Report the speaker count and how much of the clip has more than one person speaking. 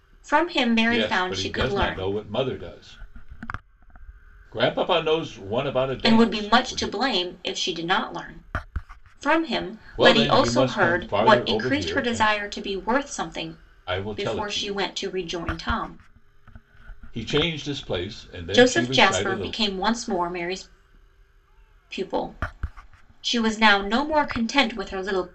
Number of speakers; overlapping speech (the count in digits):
2, about 25%